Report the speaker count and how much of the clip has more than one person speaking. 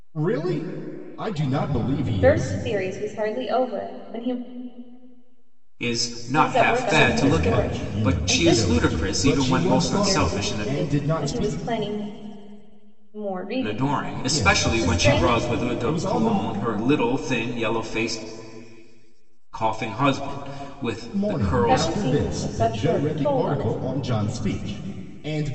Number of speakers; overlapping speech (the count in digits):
3, about 44%